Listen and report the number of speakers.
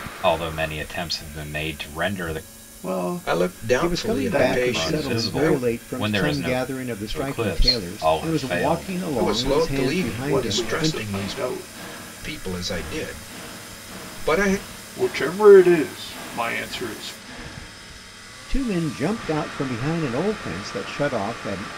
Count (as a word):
four